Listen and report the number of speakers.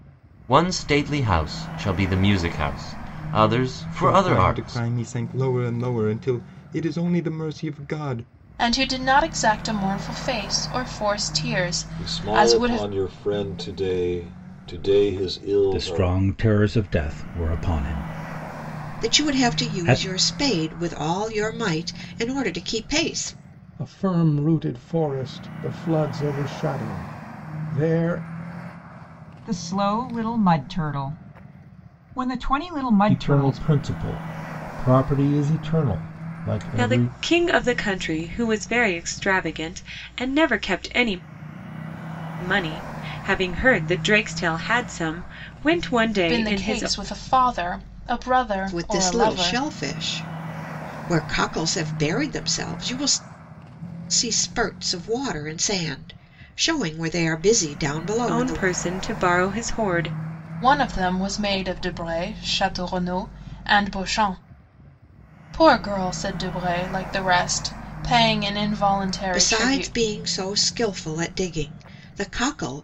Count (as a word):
ten